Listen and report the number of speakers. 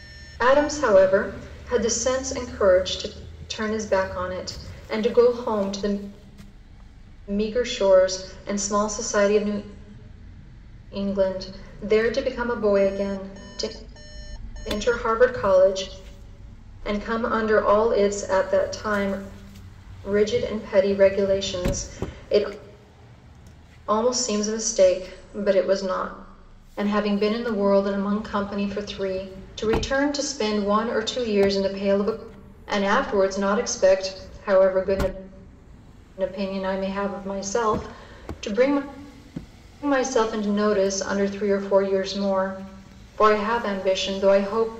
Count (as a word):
one